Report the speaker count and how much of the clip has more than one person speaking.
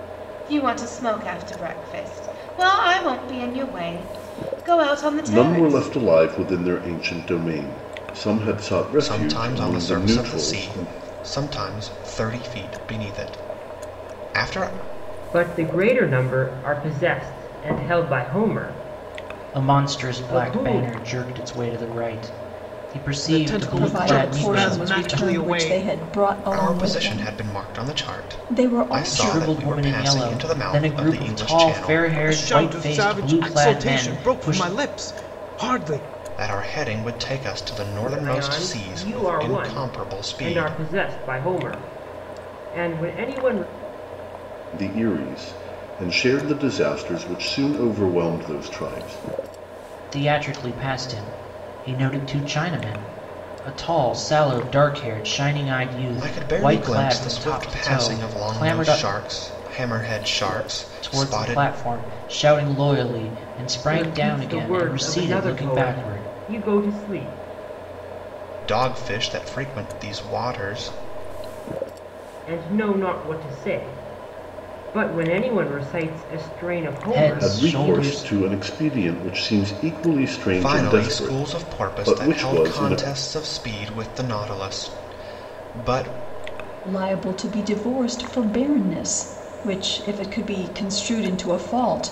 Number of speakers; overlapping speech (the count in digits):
7, about 29%